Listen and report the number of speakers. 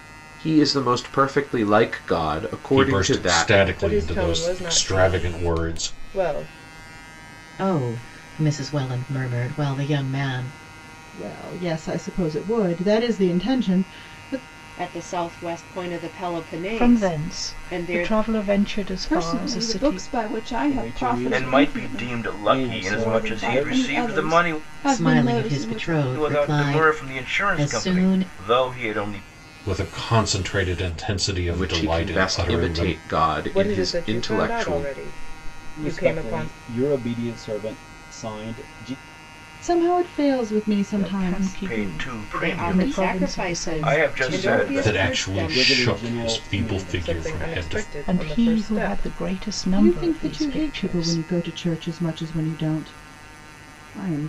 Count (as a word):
ten